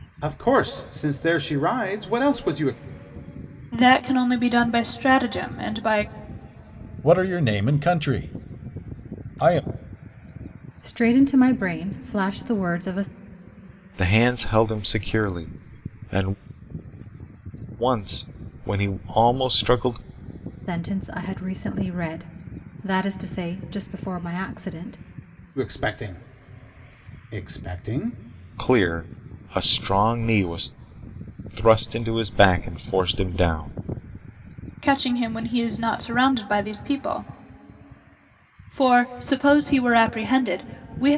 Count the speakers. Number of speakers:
5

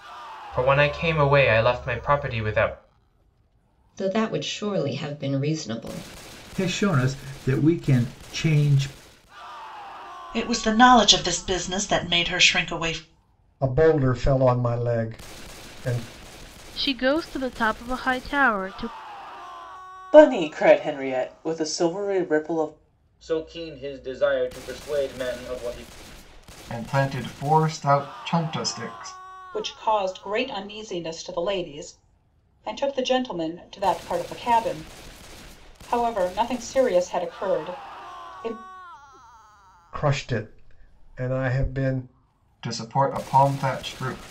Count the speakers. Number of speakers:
10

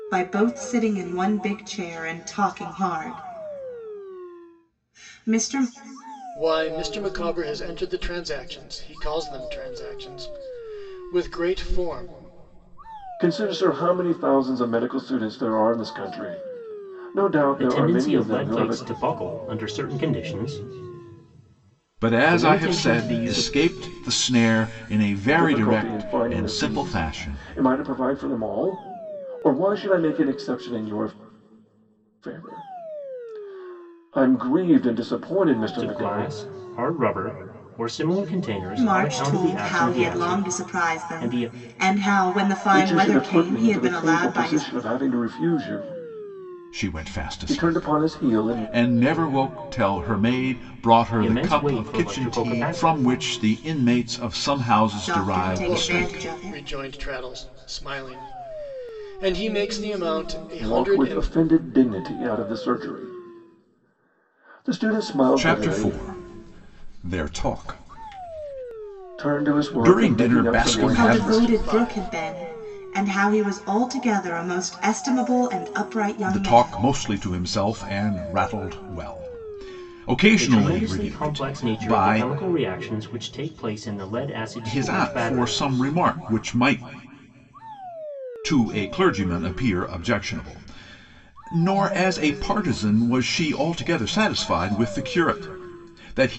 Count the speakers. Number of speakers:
5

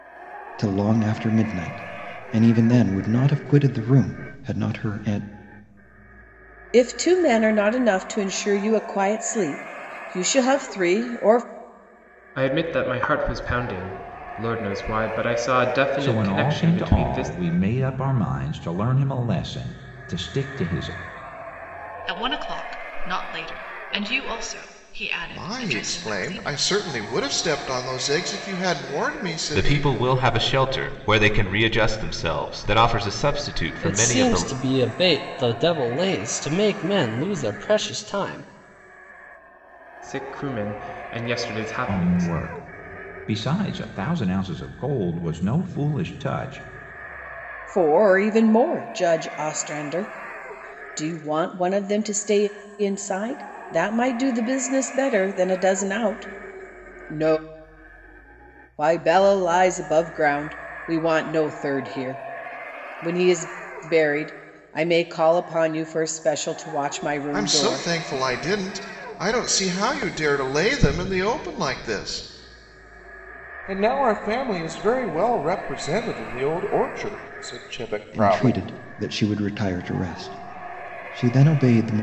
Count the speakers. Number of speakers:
8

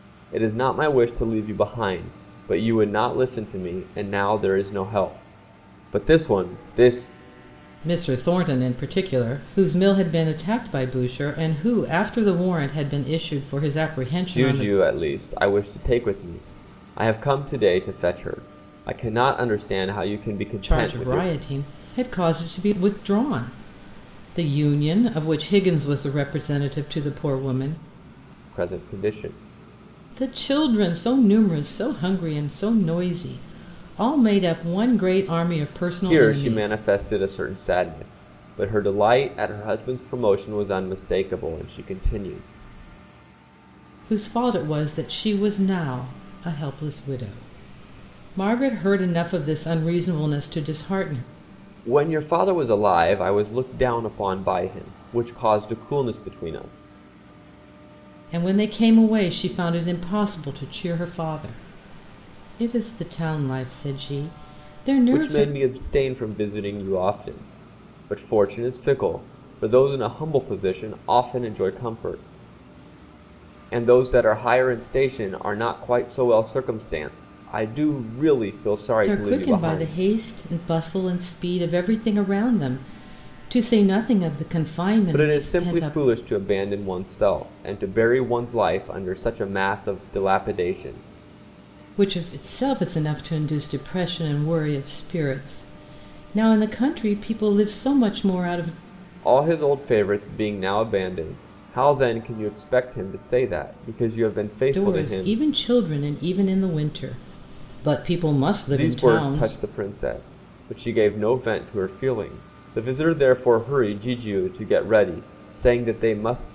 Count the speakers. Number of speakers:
2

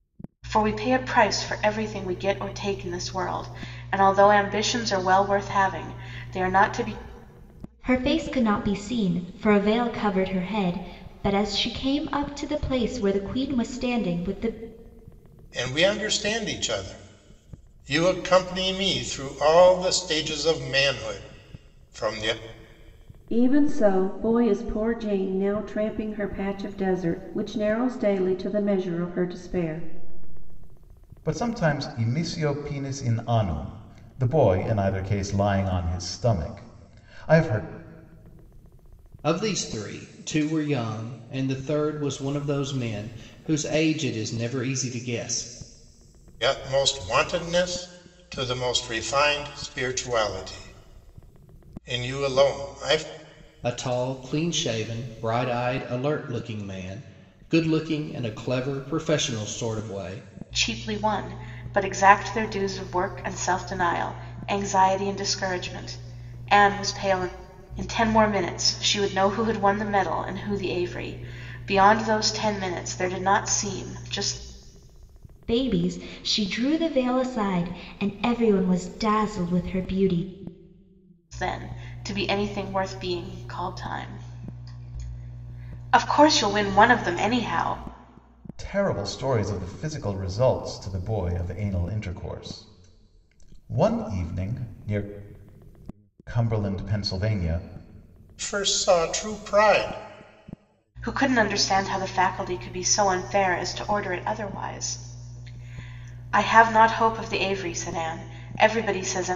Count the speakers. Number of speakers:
6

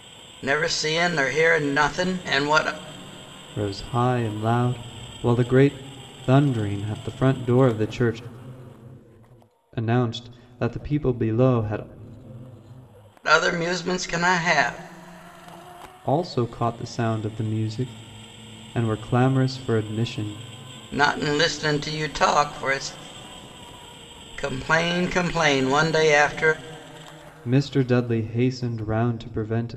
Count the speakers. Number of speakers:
2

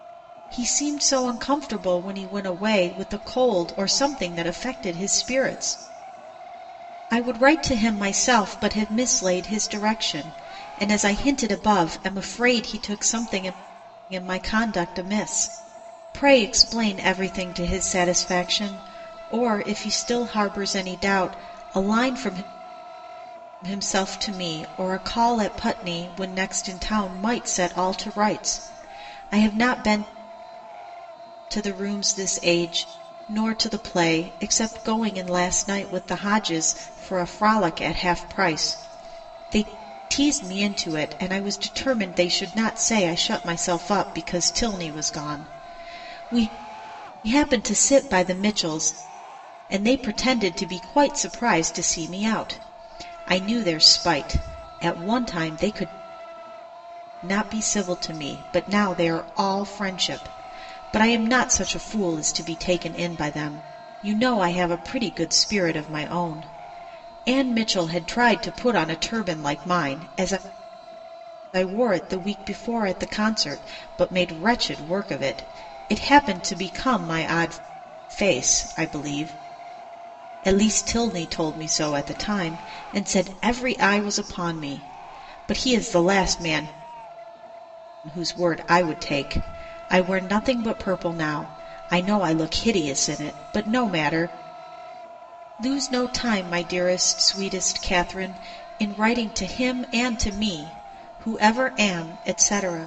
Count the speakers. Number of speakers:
1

